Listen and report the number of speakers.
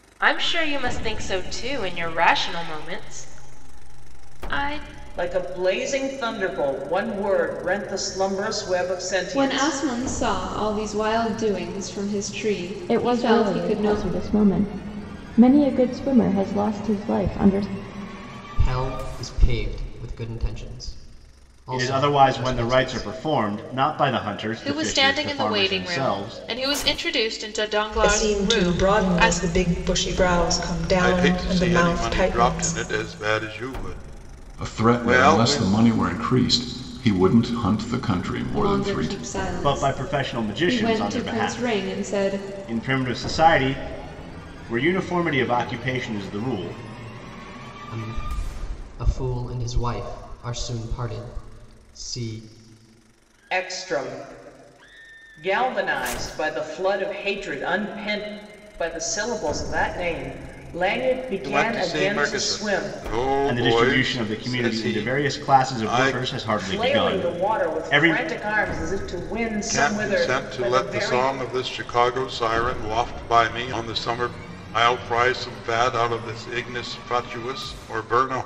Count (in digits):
10